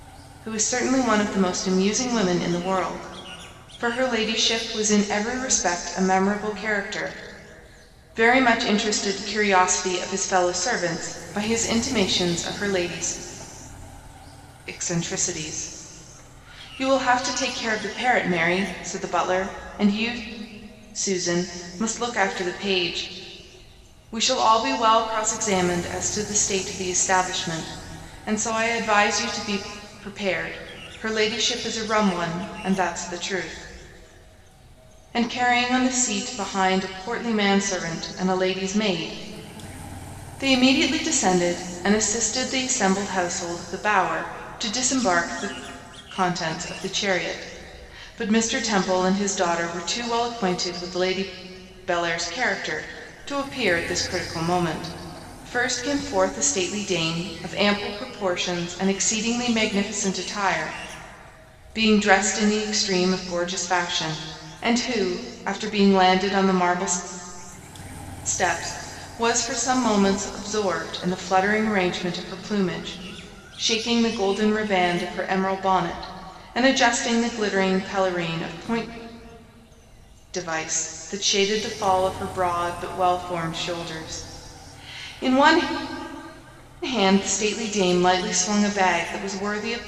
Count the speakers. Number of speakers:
one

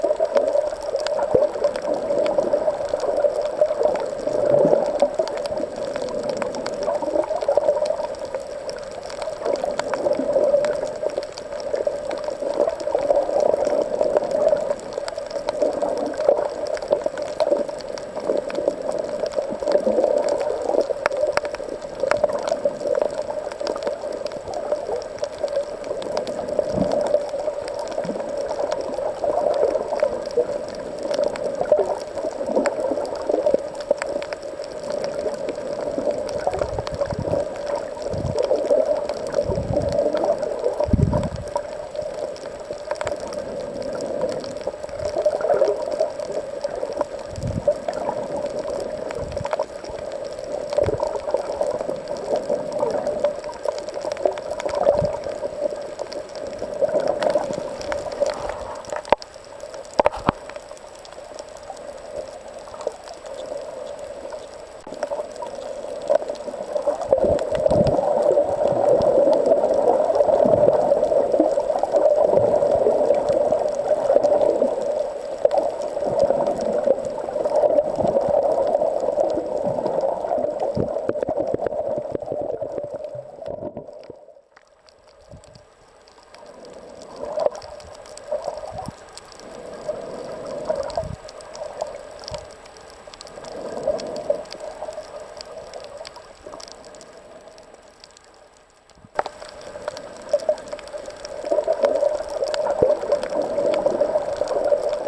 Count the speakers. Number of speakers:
zero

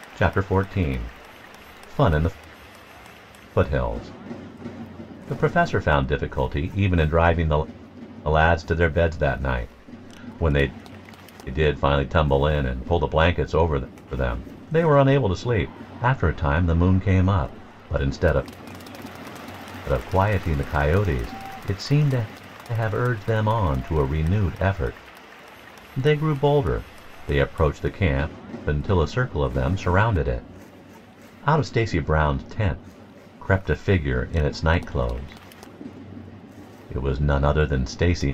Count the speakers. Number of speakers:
one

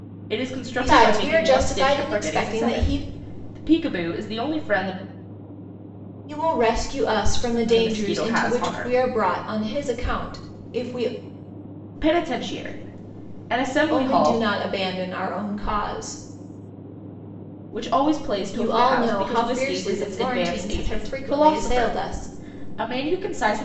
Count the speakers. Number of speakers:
two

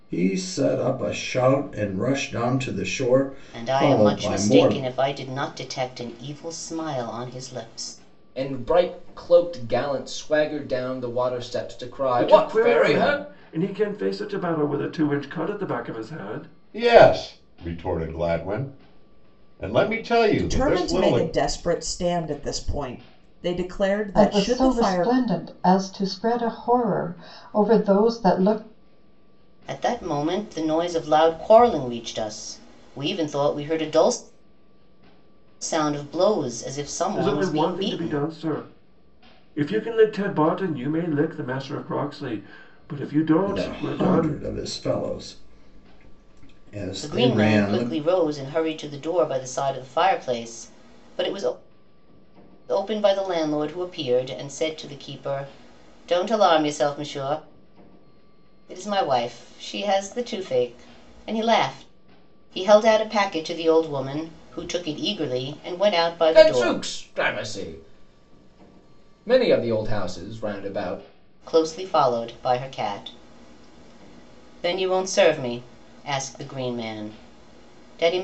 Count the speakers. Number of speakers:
seven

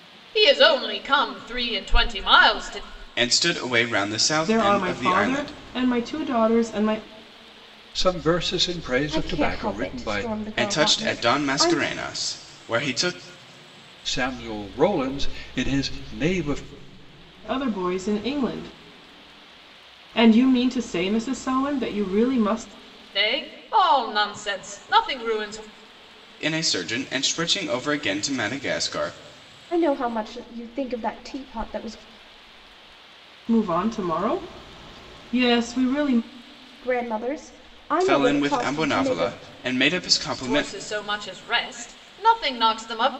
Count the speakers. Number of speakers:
five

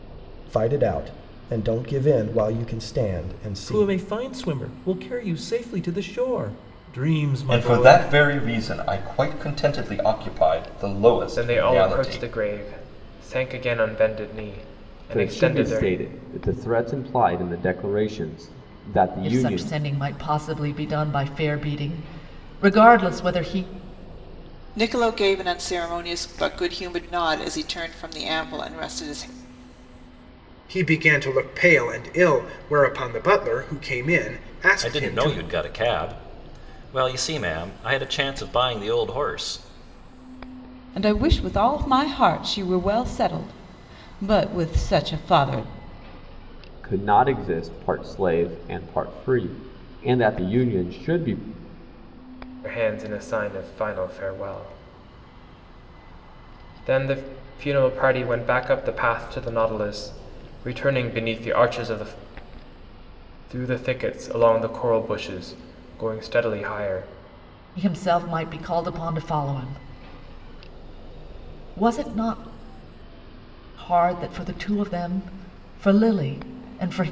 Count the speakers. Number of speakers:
ten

